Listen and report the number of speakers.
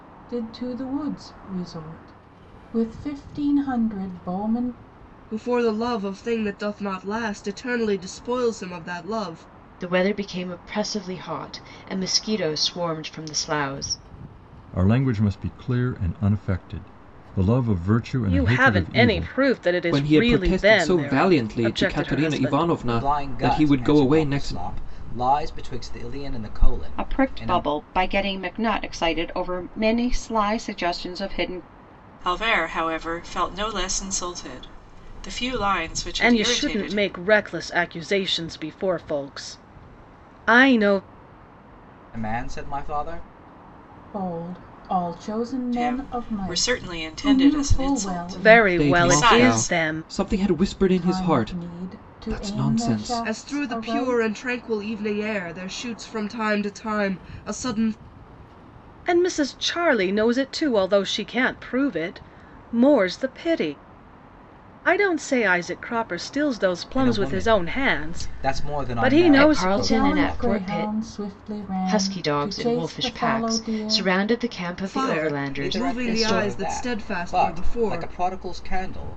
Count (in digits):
9